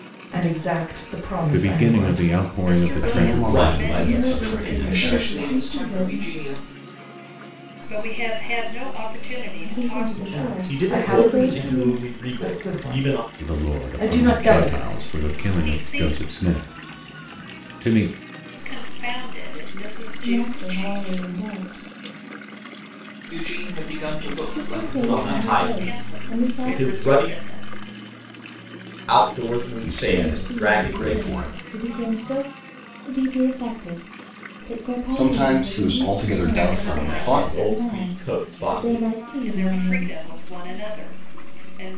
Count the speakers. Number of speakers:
7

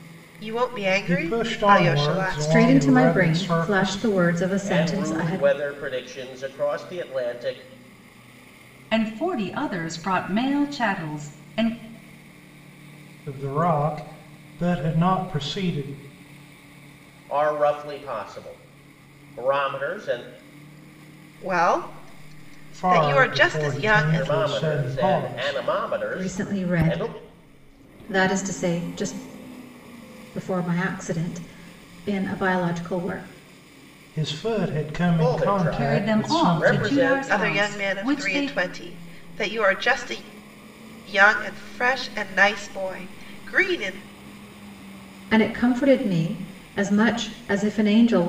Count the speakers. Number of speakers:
5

